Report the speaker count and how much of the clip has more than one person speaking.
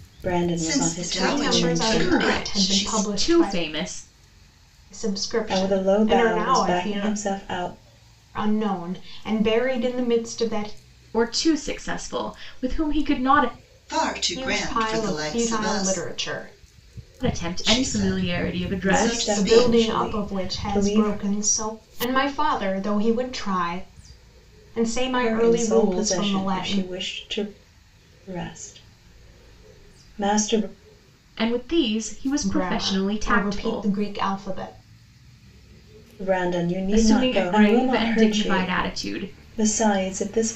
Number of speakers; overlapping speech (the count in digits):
4, about 39%